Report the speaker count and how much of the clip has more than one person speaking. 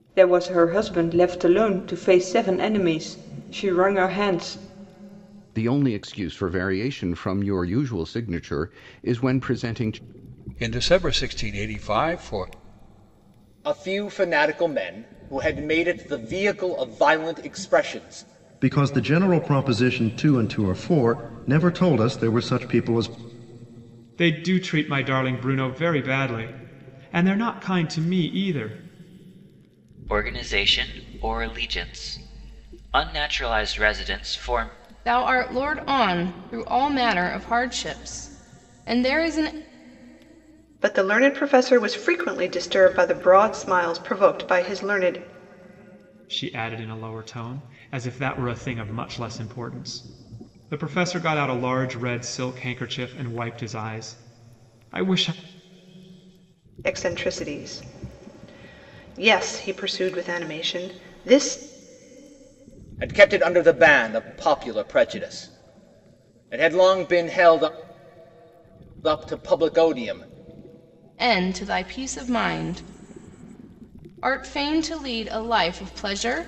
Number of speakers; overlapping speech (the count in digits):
9, no overlap